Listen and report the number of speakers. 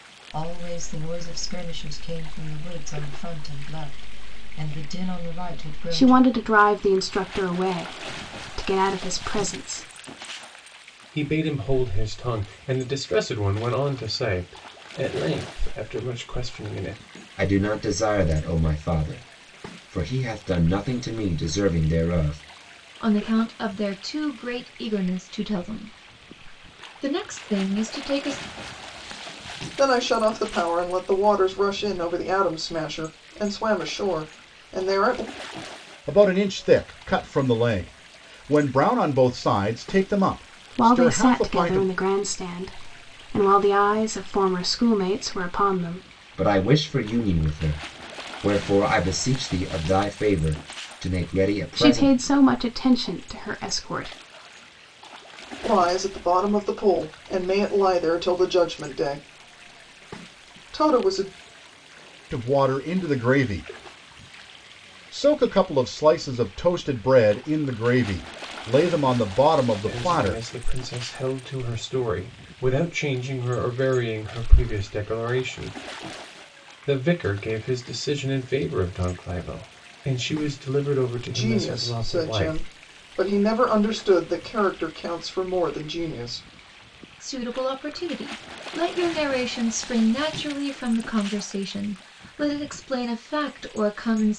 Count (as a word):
seven